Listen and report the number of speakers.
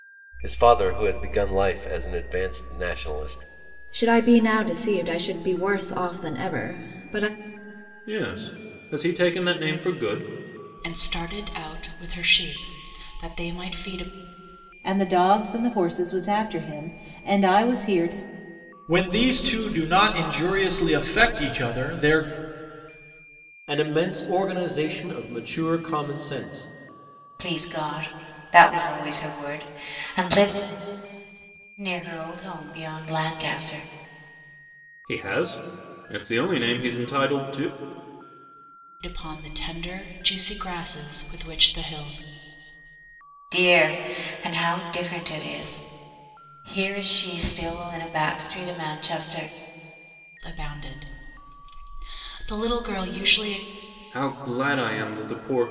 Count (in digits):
8